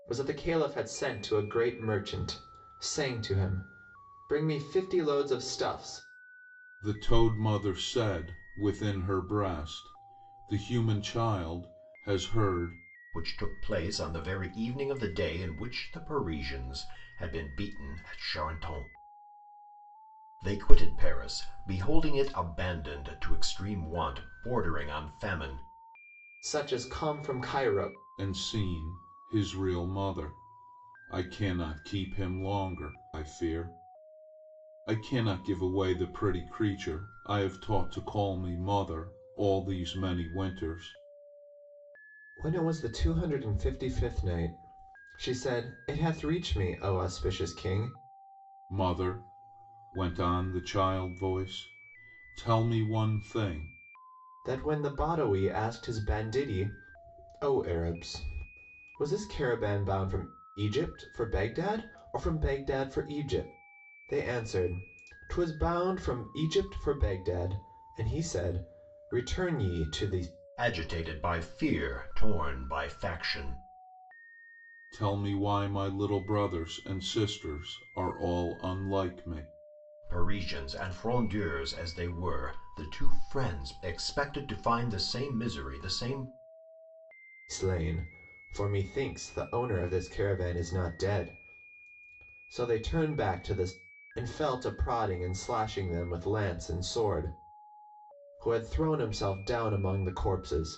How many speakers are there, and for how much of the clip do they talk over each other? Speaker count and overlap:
3, no overlap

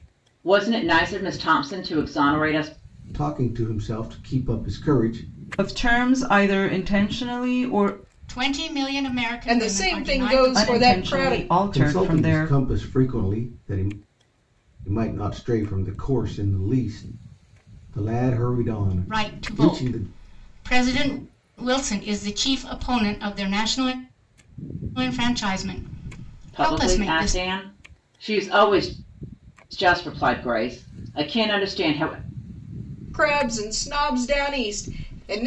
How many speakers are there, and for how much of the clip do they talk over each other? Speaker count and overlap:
5, about 14%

